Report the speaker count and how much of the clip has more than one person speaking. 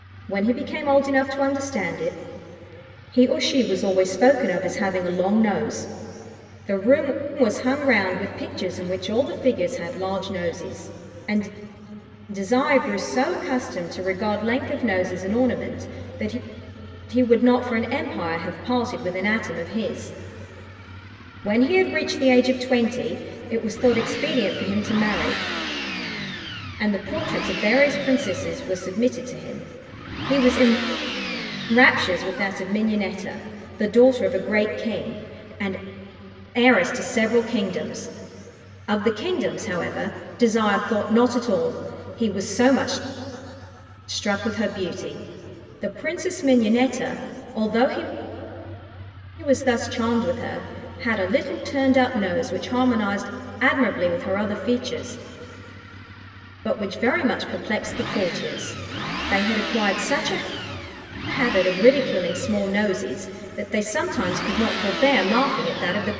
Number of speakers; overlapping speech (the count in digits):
1, no overlap